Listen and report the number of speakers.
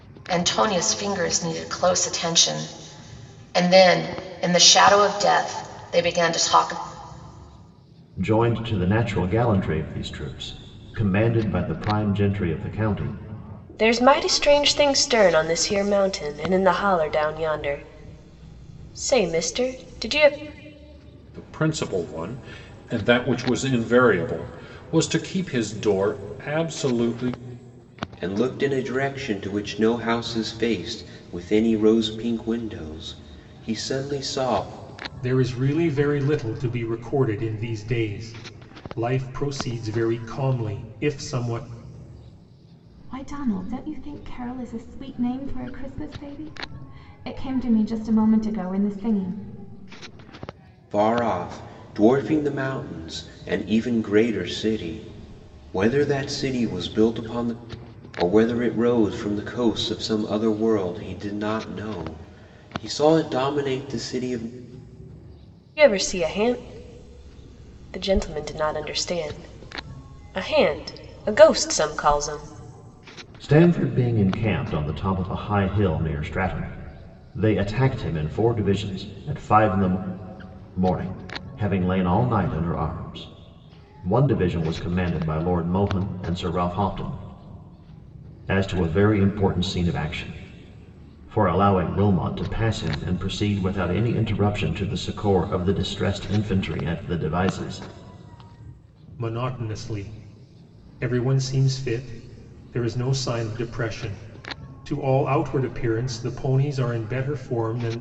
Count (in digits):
7